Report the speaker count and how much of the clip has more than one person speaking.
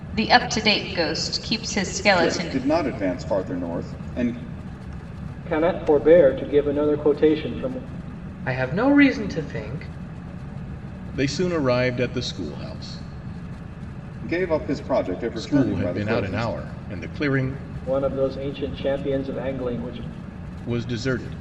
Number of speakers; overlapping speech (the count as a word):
five, about 8%